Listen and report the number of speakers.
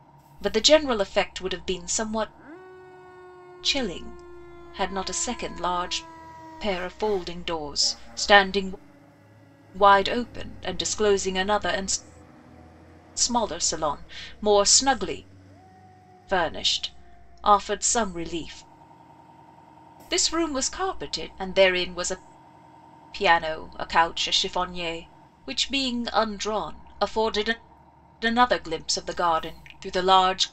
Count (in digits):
1